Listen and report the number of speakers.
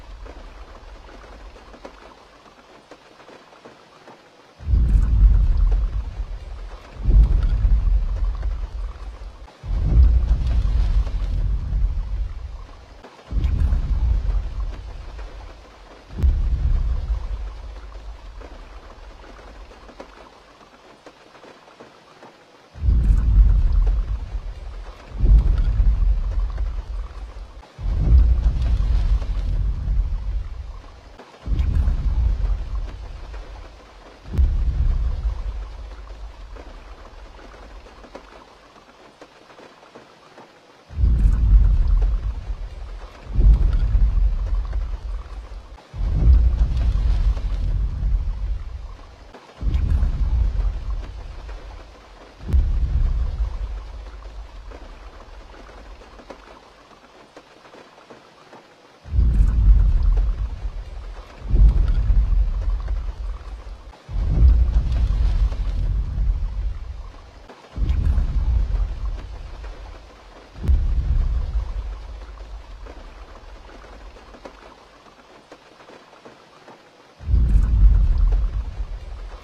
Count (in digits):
0